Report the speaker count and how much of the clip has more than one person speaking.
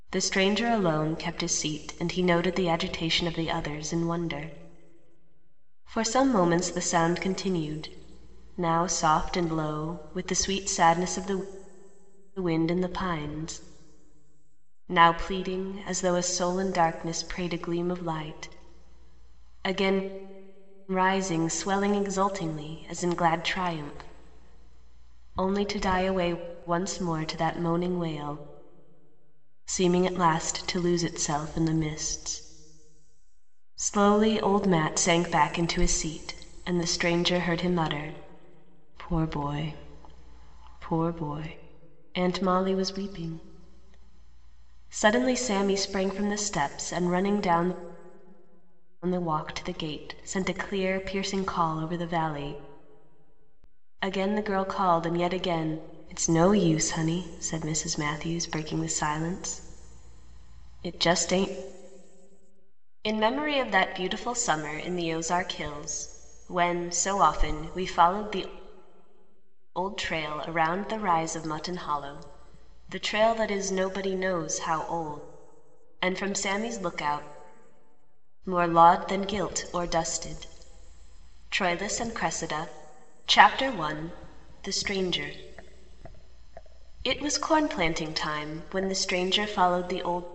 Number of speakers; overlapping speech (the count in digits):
1, no overlap